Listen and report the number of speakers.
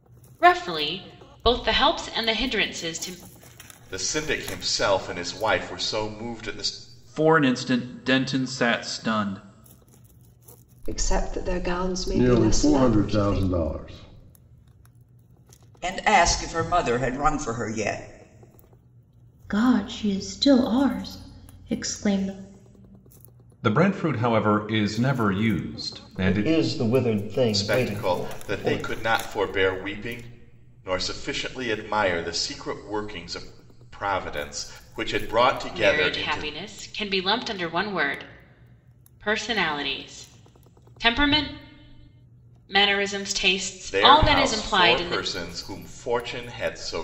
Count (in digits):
9